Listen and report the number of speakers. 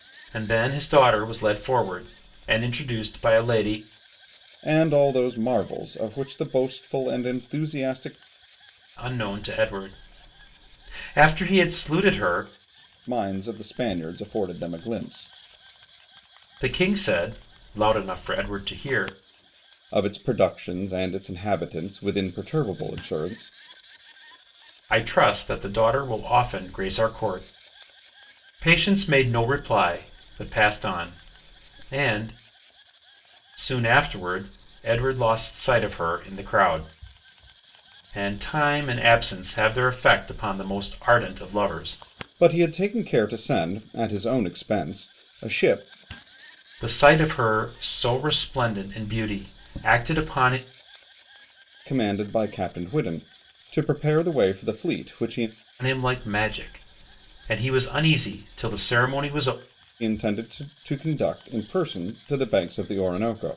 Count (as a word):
two